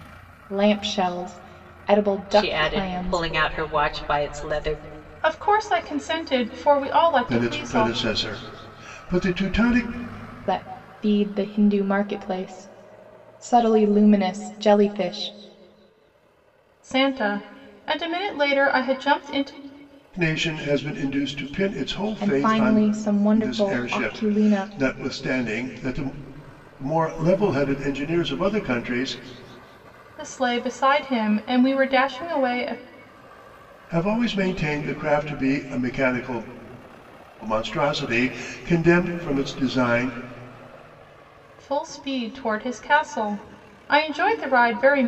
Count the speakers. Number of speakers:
4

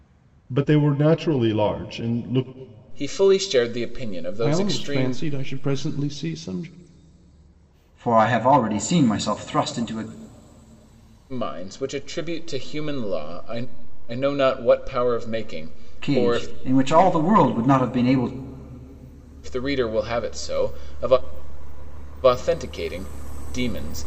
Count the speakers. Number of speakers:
4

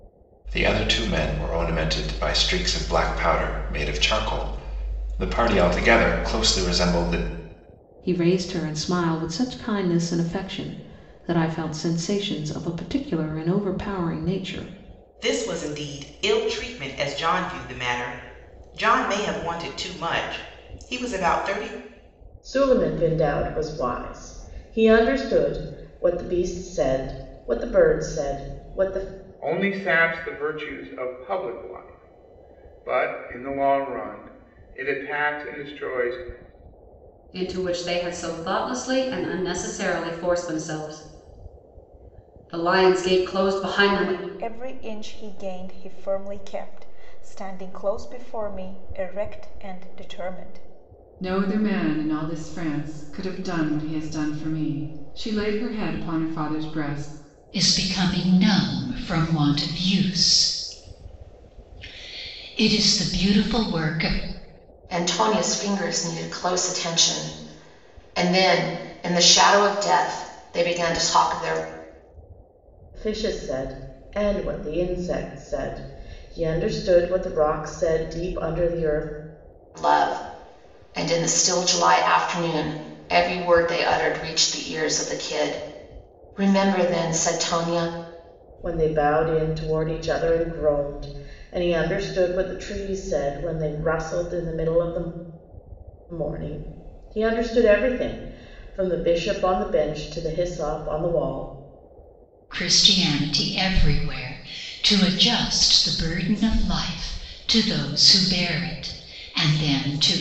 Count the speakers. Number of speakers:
10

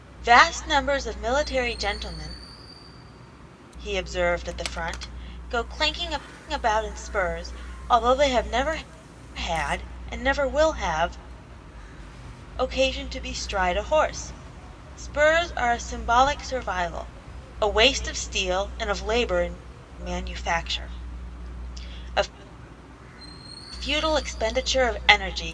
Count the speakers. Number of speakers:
1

